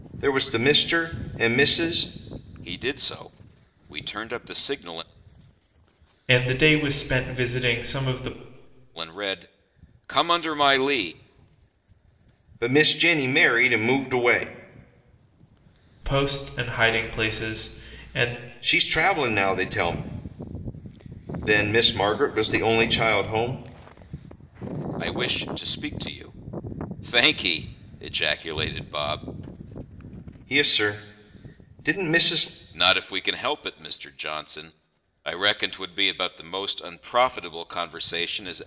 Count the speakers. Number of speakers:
three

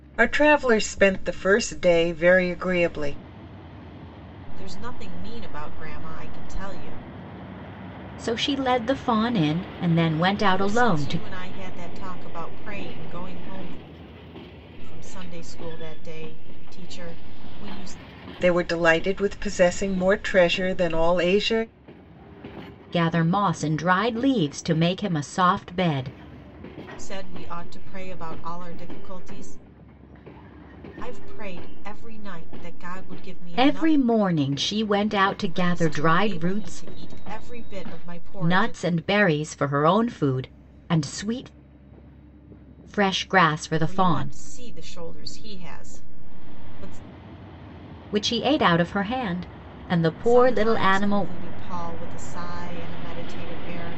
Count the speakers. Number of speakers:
three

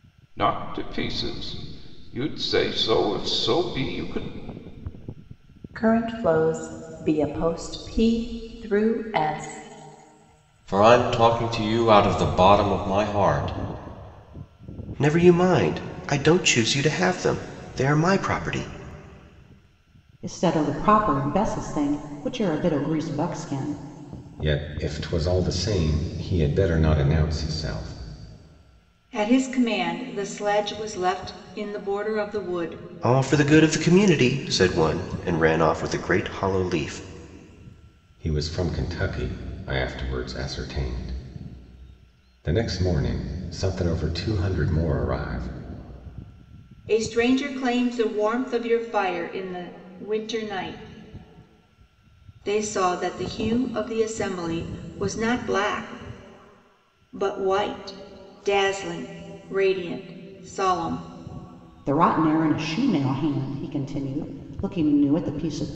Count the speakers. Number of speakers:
seven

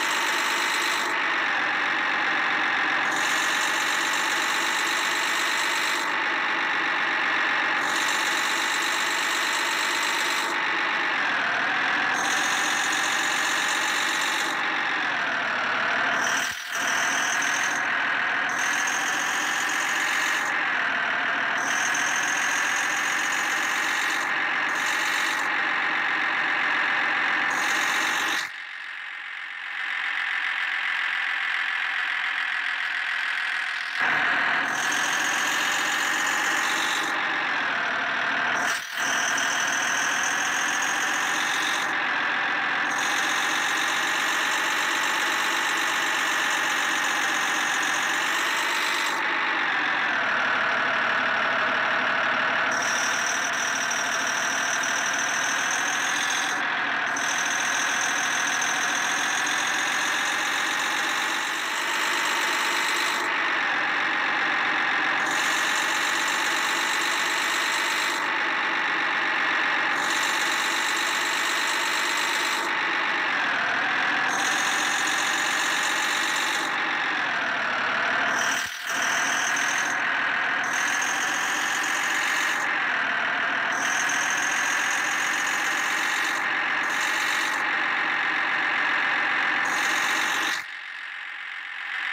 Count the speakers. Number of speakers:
zero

